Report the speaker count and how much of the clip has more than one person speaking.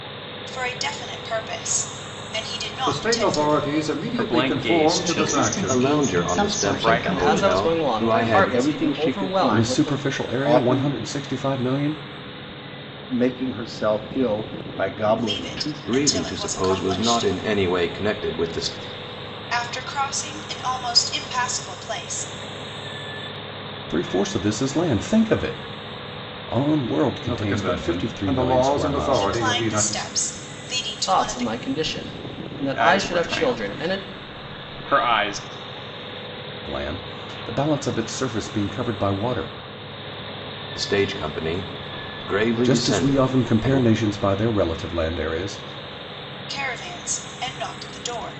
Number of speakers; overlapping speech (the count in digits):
8, about 32%